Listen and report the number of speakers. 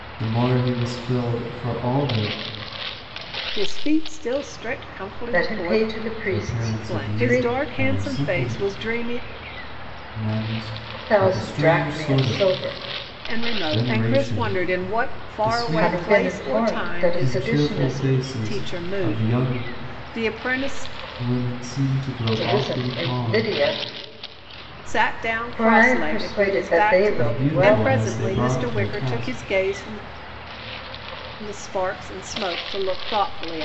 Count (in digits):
3